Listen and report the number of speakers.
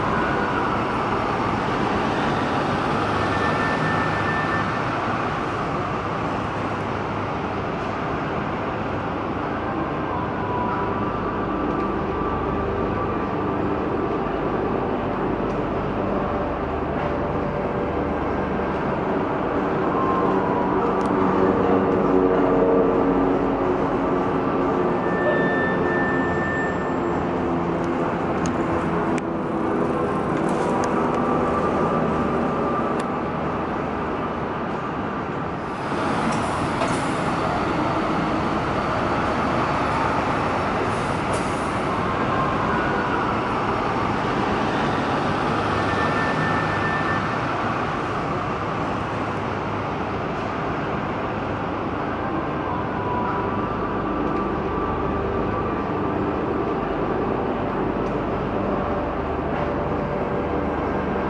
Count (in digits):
0